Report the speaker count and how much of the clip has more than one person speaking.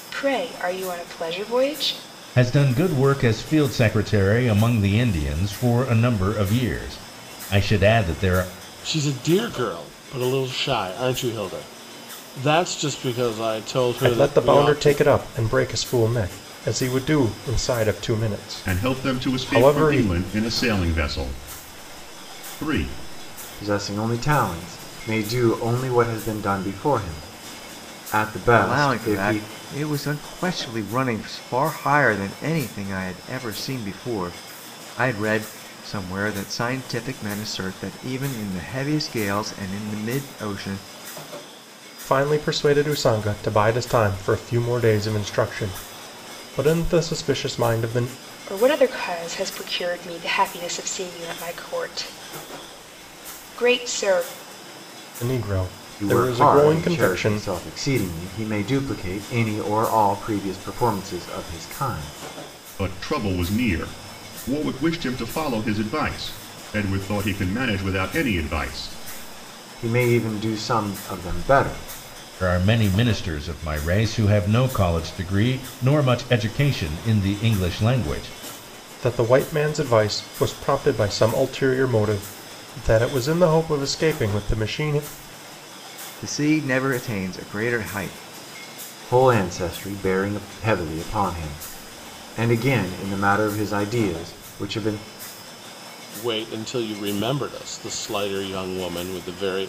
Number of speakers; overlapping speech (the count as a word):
seven, about 5%